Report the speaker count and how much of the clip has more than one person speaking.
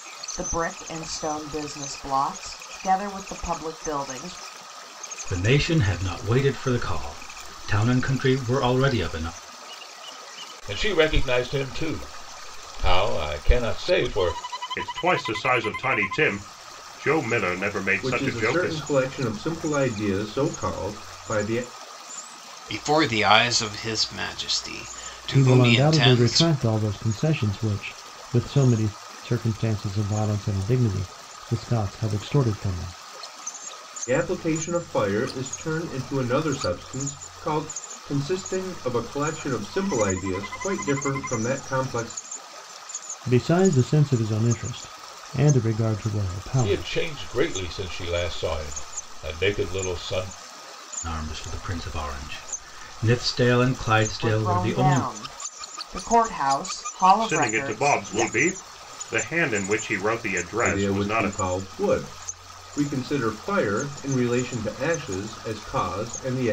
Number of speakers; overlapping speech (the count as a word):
seven, about 8%